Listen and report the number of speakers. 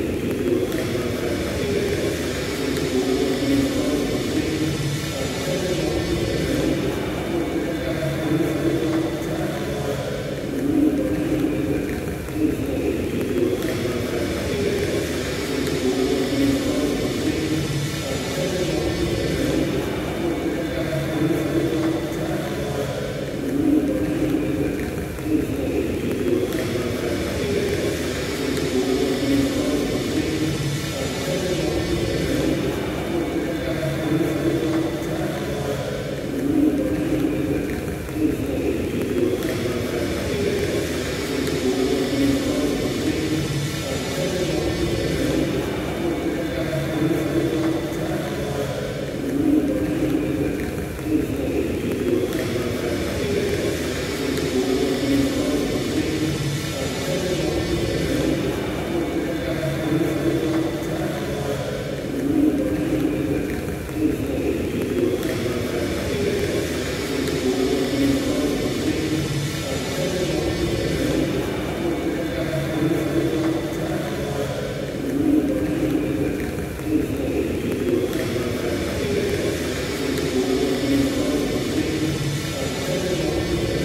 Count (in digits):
0